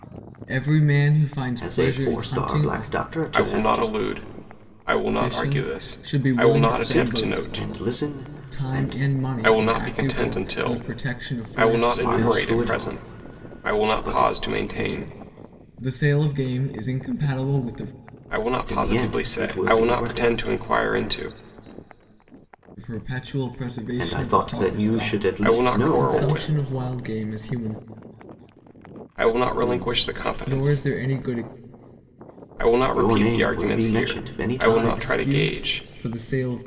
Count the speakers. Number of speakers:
3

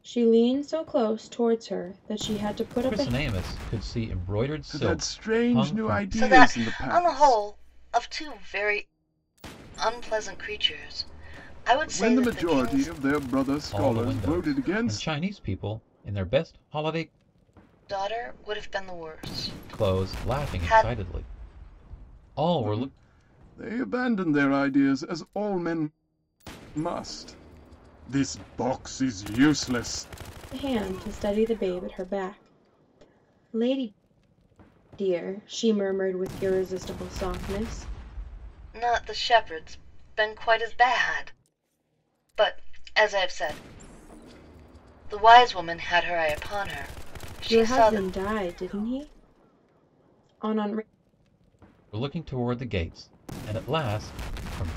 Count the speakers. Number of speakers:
4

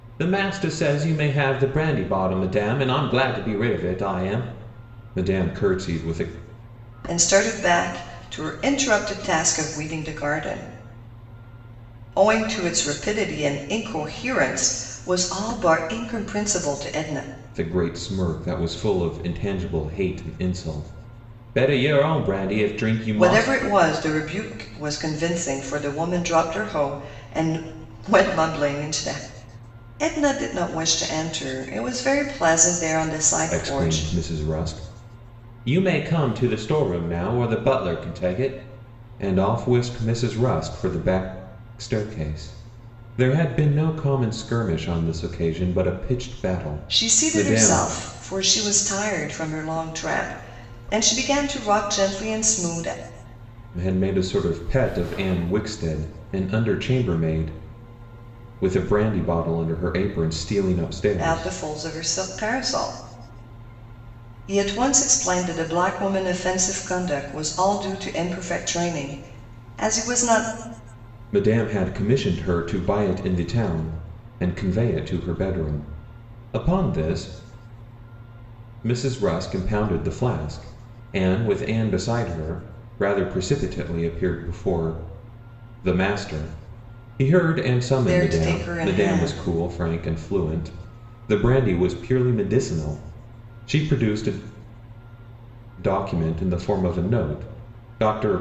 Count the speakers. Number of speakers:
2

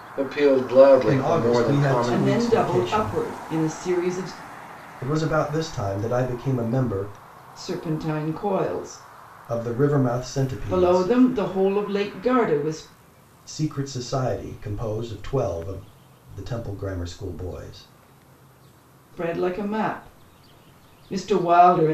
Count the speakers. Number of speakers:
3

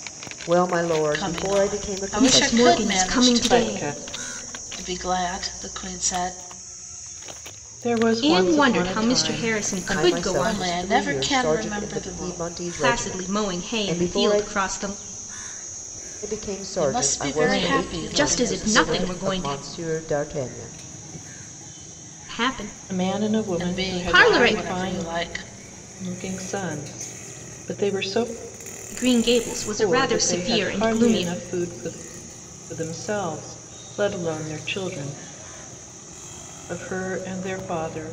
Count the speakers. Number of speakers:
4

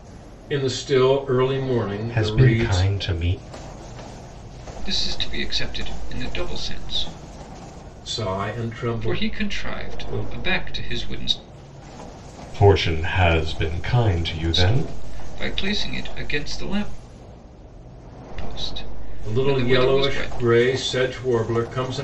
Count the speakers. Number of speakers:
3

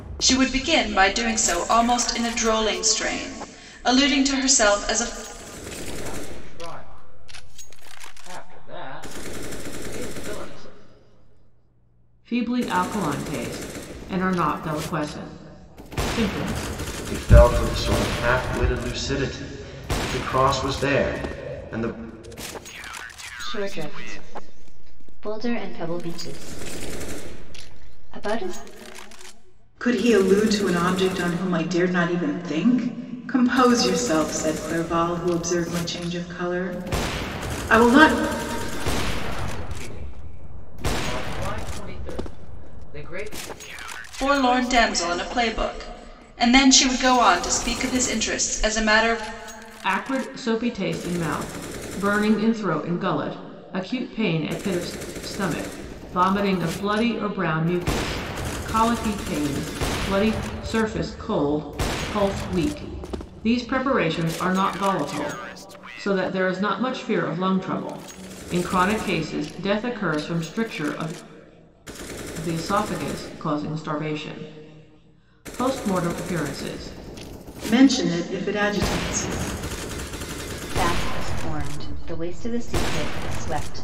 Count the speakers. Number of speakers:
6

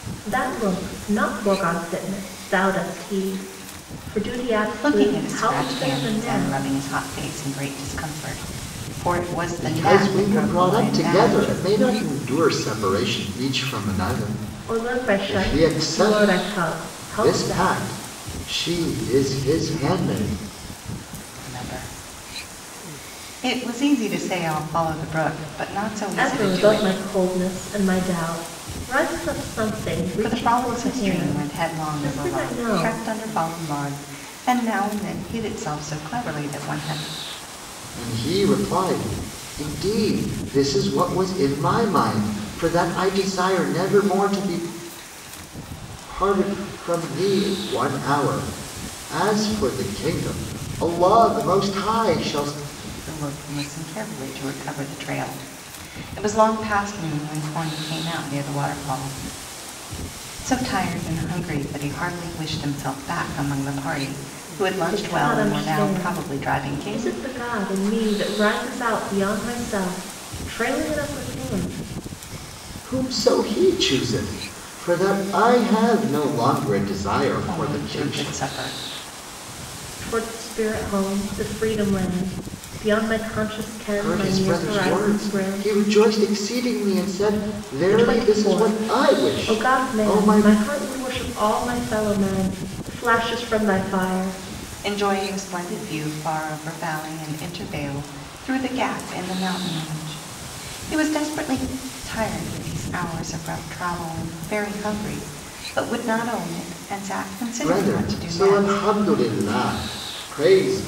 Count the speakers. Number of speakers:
3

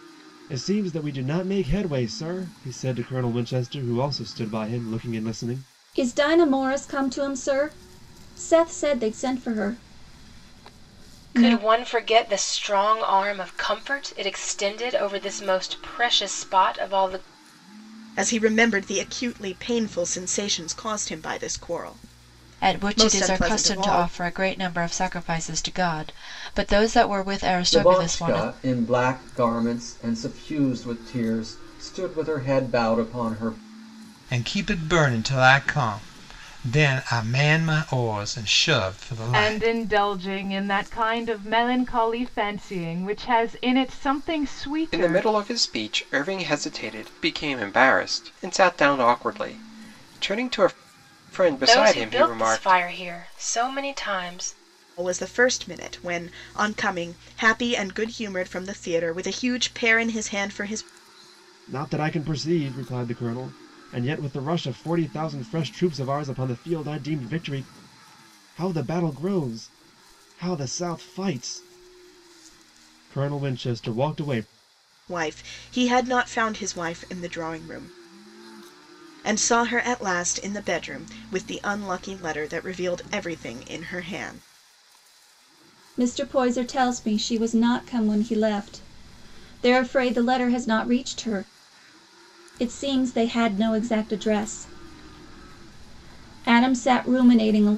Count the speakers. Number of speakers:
9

